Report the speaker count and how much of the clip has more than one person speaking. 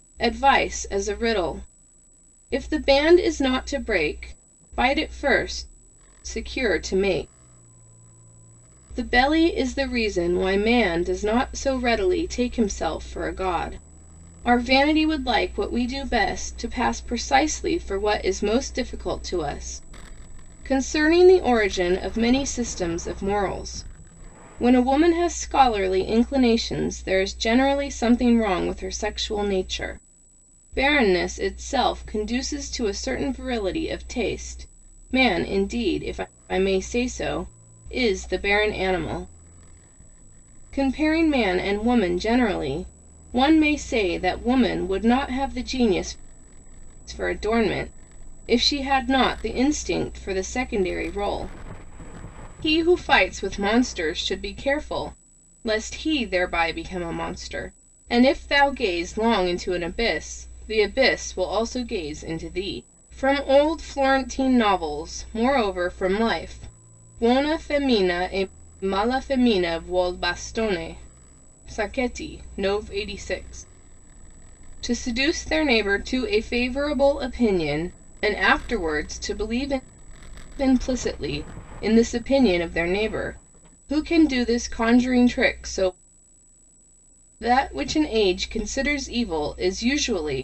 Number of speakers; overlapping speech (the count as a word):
one, no overlap